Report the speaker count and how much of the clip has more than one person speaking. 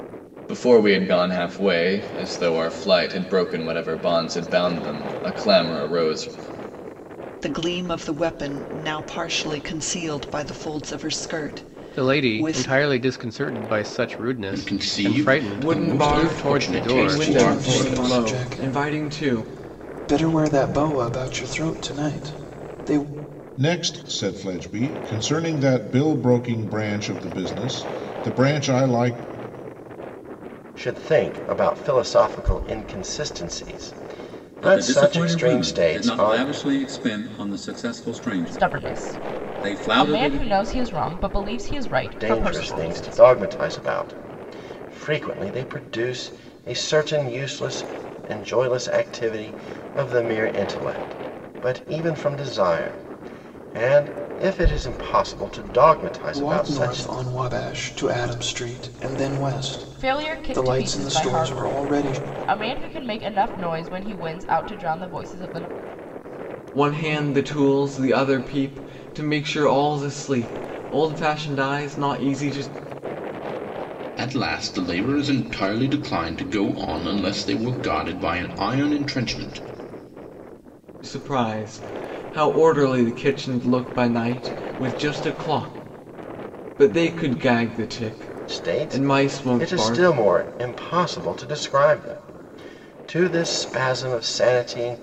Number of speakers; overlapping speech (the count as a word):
ten, about 16%